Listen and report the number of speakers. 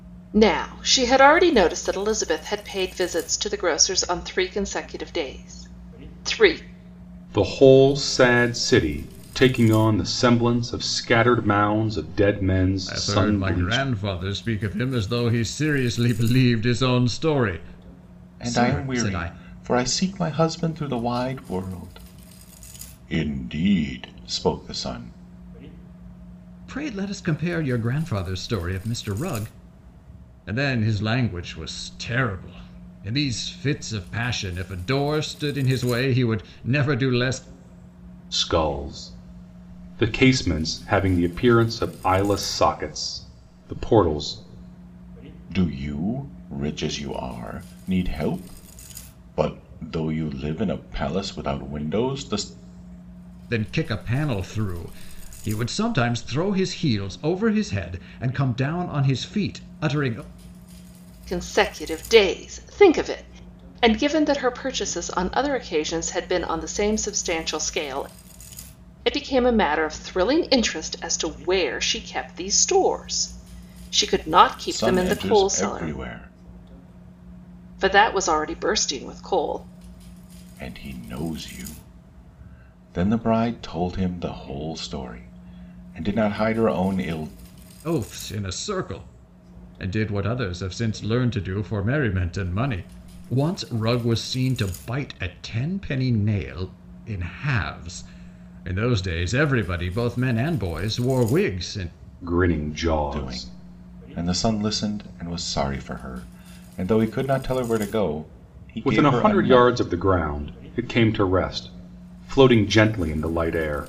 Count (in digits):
4